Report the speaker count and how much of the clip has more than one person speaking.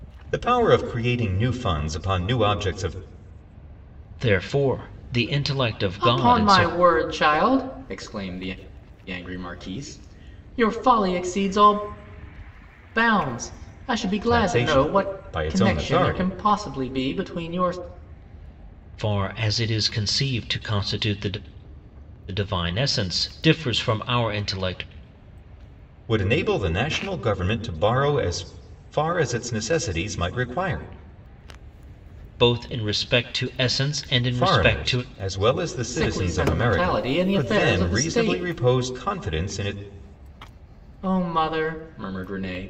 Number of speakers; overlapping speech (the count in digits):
3, about 13%